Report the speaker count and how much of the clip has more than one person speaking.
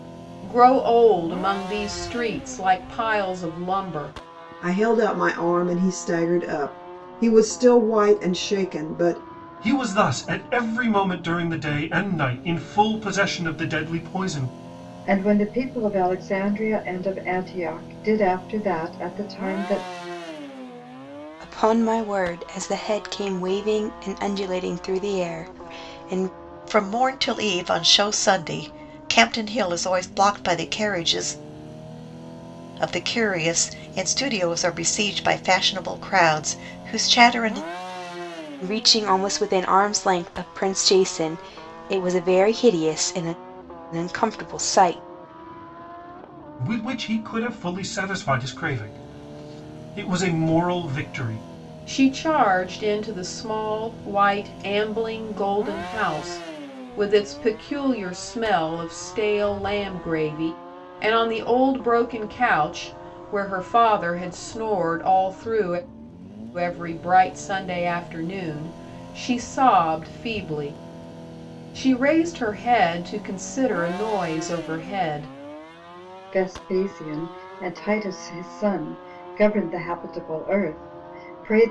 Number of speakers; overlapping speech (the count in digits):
6, no overlap